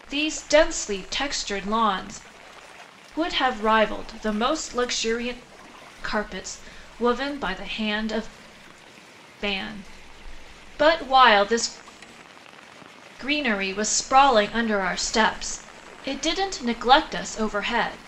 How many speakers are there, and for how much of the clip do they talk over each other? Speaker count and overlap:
1, no overlap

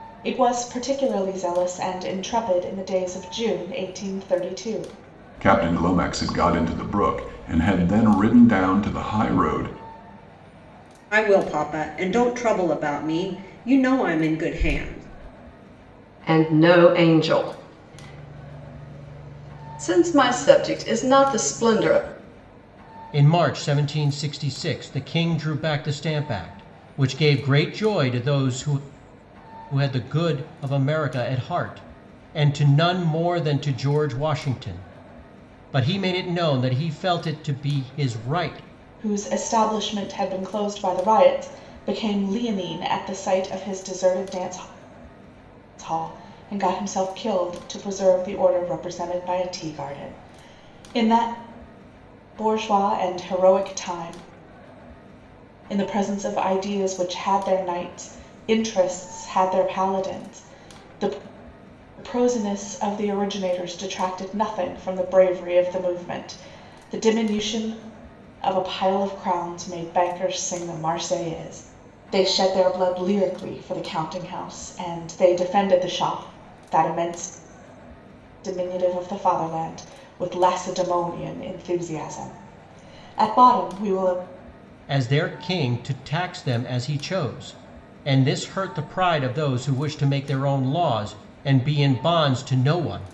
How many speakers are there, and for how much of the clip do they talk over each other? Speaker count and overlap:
5, no overlap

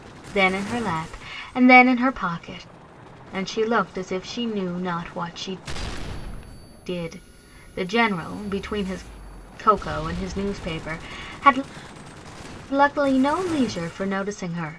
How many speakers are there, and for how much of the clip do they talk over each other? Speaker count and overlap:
1, no overlap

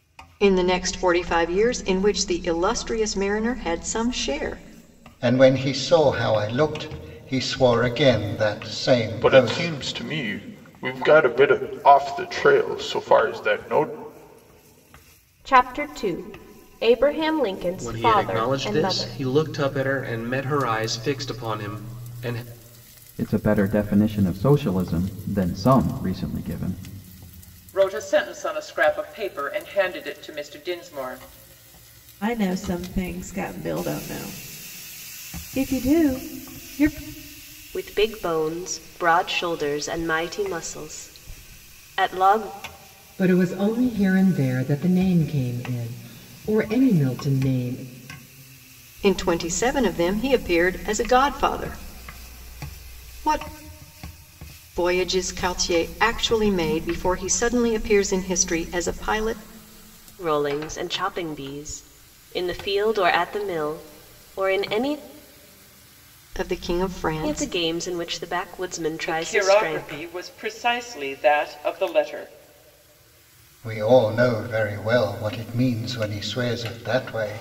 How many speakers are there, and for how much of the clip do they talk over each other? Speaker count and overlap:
10, about 5%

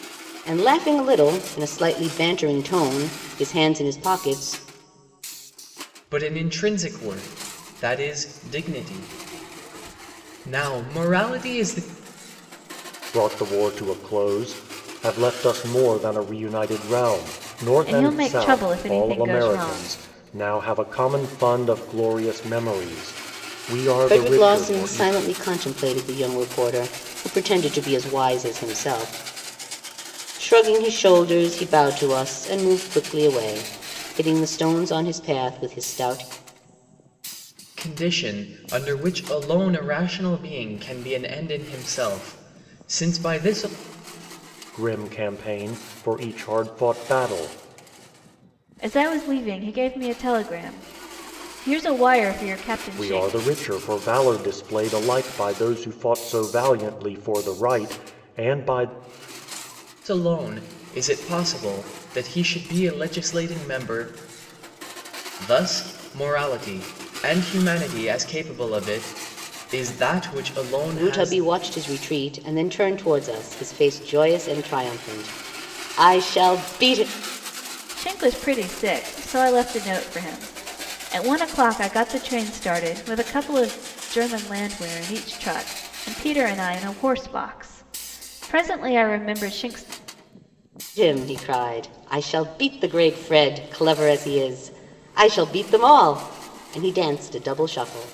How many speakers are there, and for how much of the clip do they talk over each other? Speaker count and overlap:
4, about 5%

